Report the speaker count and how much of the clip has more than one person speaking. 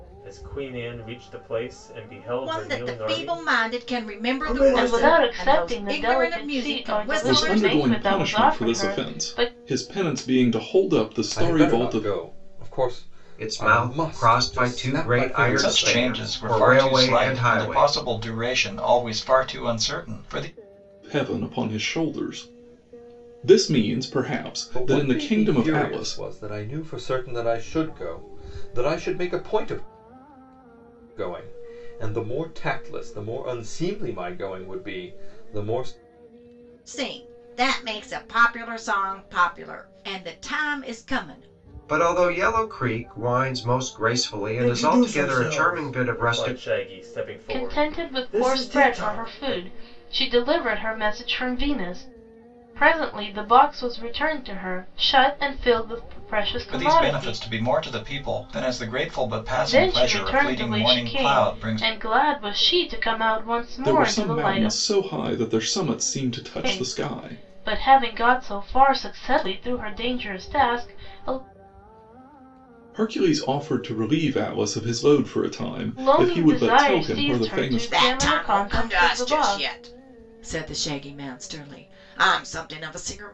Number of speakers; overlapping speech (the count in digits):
7, about 32%